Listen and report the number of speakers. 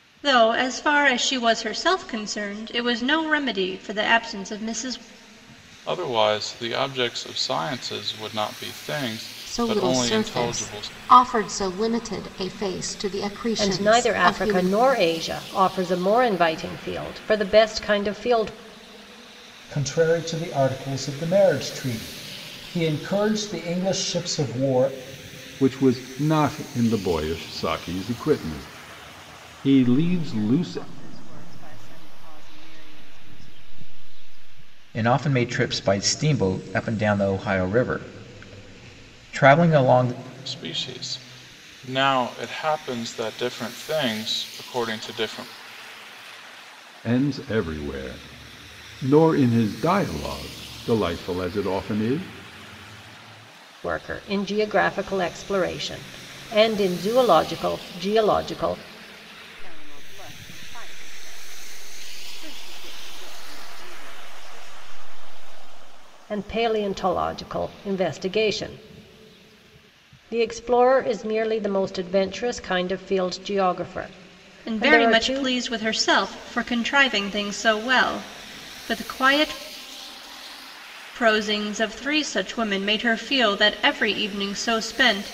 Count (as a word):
eight